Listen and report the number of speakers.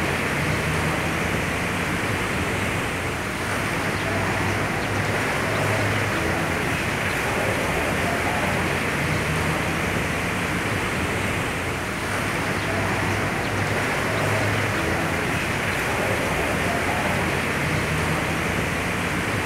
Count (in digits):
0